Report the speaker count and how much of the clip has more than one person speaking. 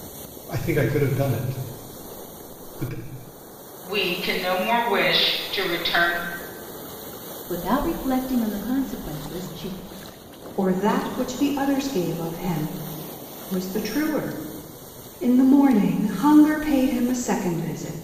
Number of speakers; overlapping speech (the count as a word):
four, no overlap